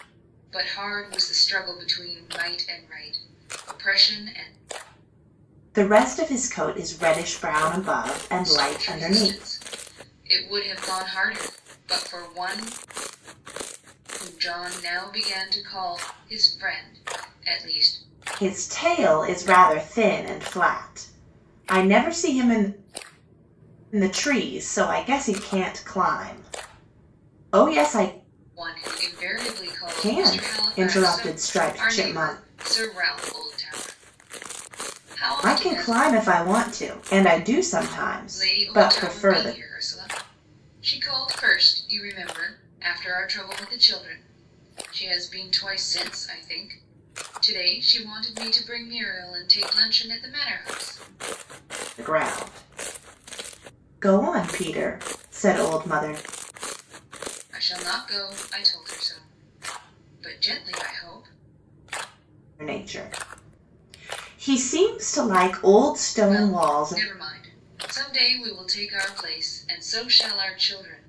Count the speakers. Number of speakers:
2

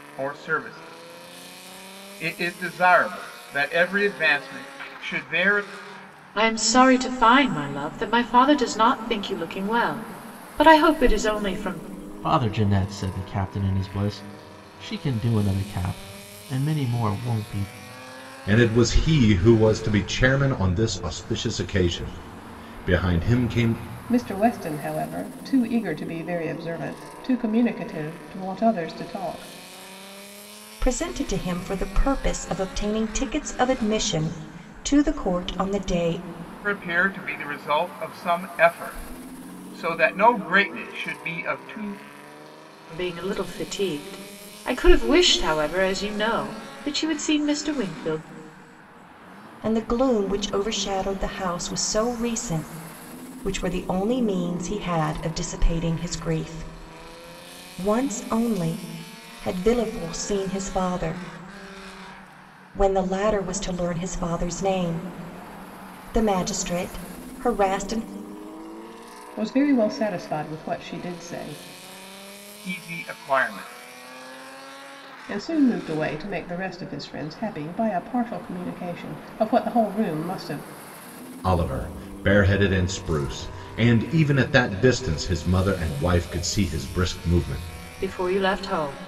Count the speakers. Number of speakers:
6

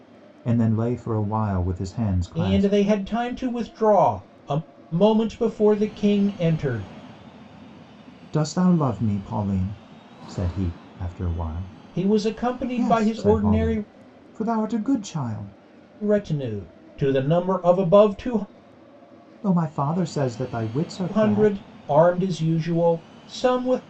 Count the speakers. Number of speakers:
2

